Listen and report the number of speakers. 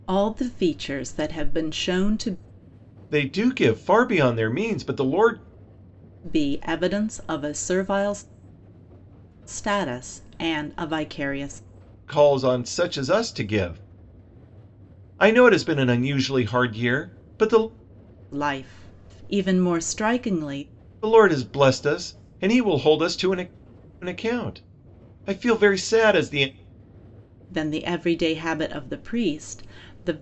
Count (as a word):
two